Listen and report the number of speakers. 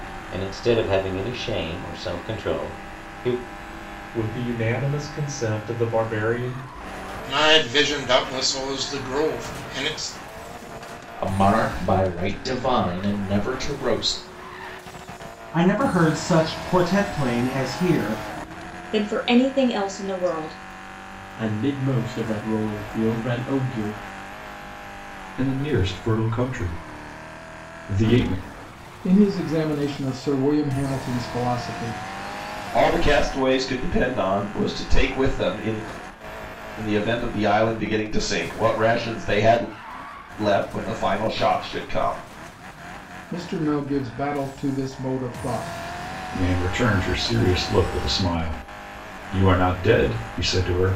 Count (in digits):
10